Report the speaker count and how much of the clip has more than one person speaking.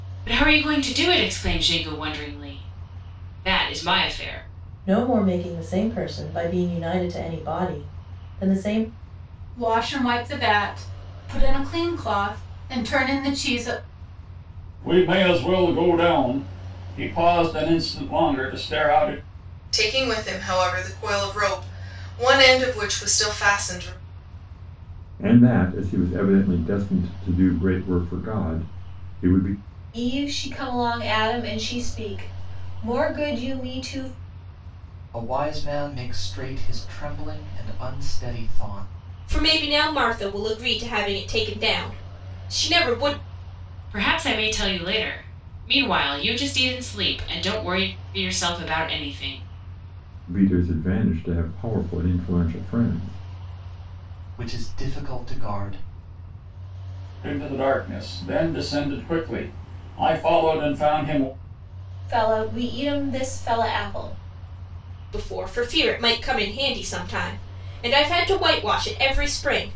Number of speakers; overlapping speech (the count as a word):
nine, no overlap